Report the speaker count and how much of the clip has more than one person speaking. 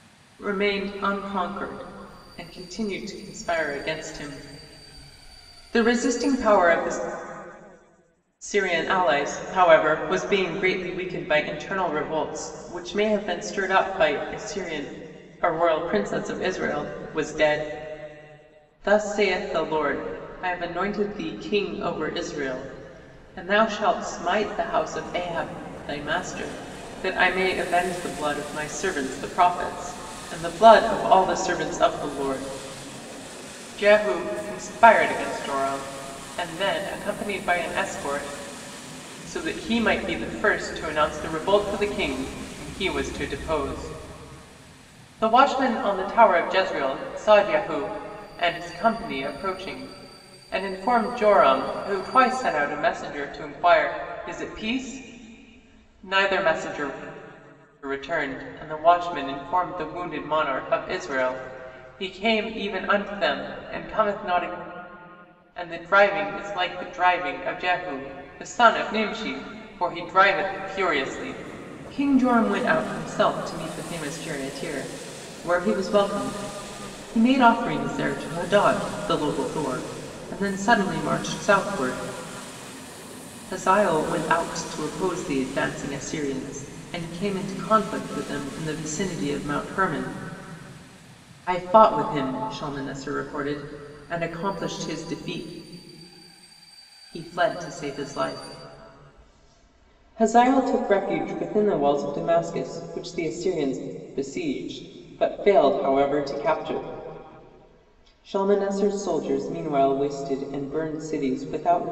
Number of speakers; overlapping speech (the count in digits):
1, no overlap